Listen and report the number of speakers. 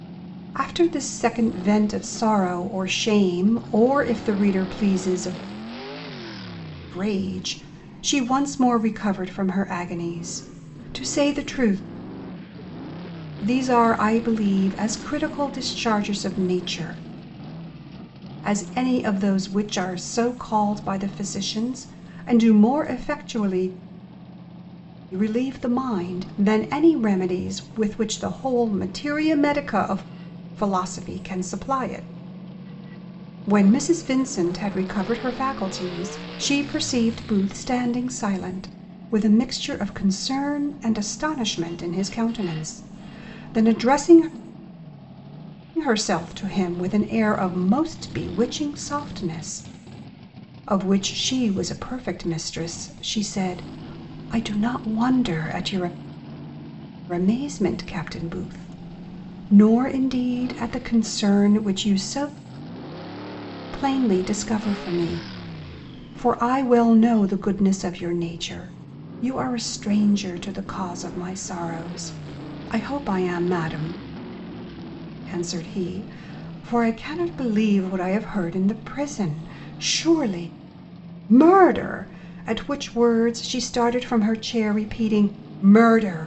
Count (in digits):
1